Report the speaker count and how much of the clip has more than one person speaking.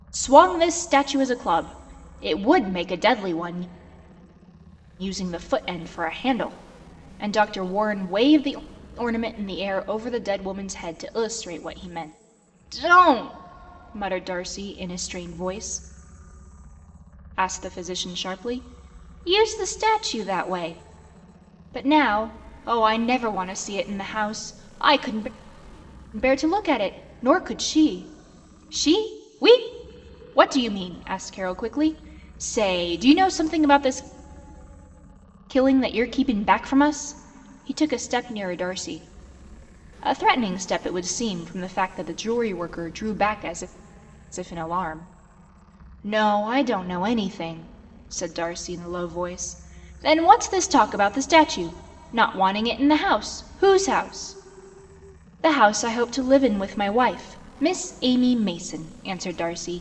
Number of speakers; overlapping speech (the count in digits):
1, no overlap